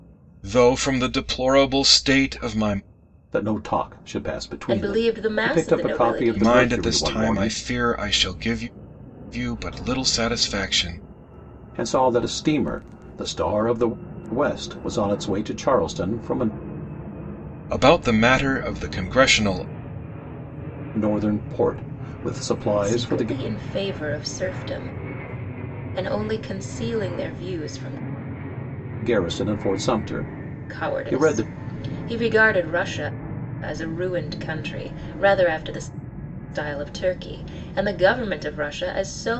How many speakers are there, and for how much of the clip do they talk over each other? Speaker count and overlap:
three, about 10%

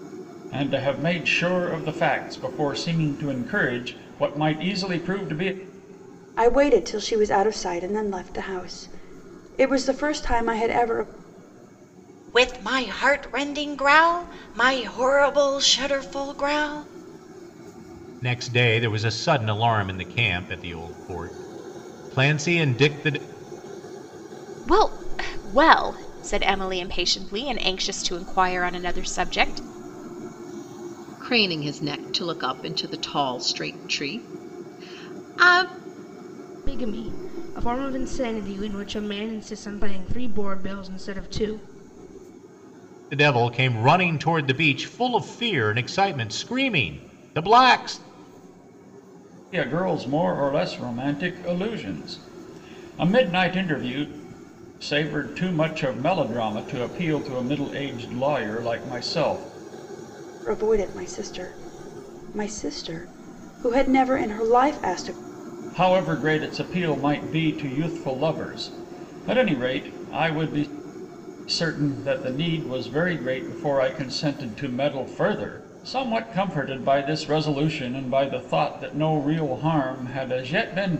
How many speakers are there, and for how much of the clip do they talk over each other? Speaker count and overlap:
seven, no overlap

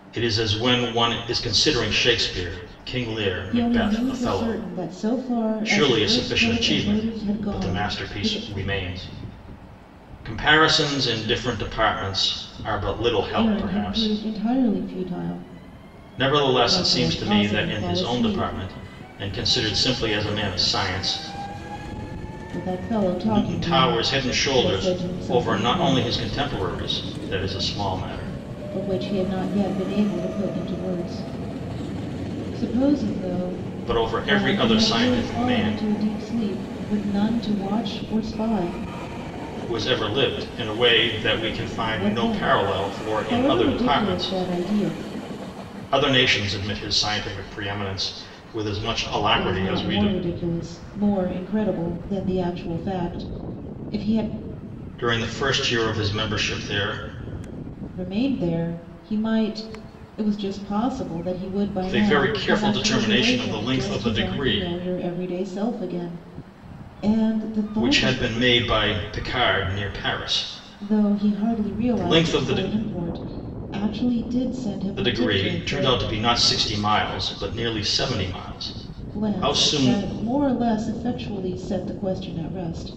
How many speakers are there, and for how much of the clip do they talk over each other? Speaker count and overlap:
two, about 26%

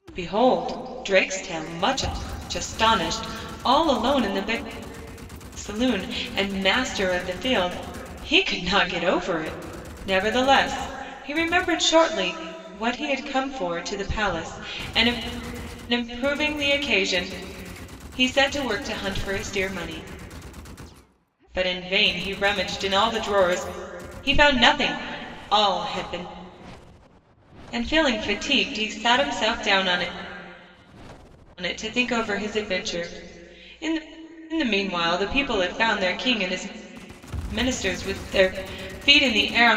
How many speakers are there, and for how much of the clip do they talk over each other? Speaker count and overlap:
one, no overlap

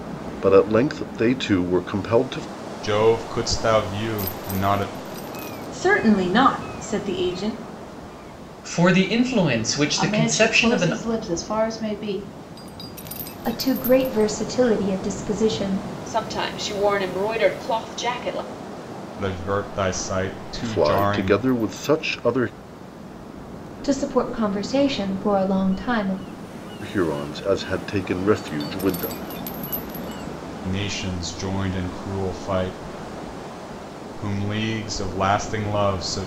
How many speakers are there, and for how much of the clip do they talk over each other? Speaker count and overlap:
seven, about 5%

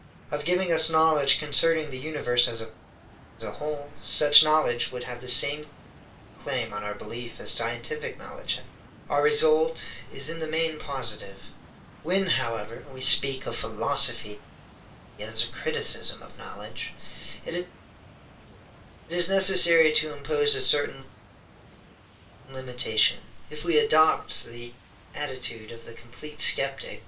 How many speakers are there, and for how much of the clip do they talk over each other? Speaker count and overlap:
one, no overlap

